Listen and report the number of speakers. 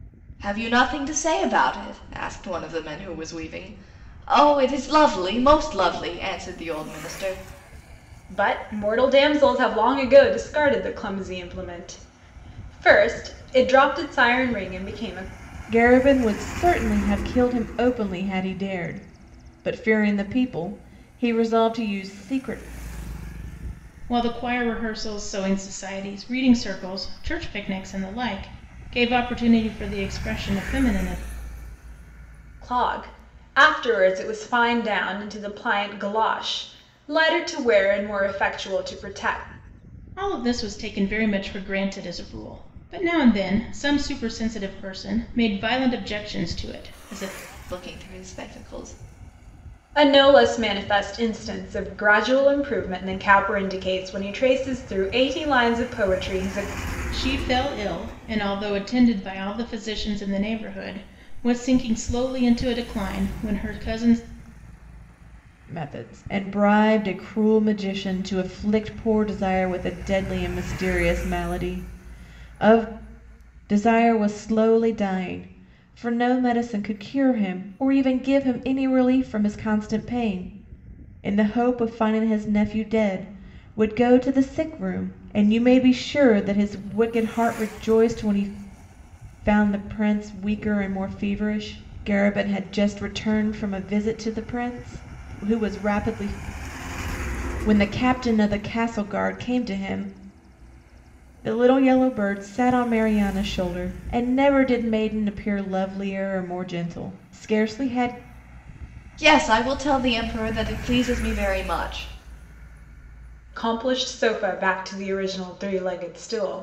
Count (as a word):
four